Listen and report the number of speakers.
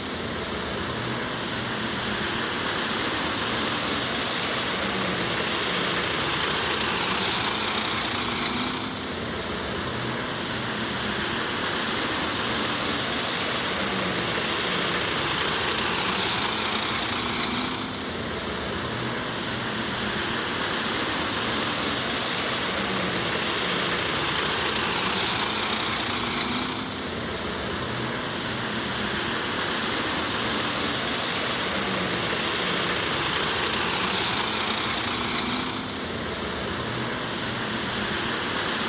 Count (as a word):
zero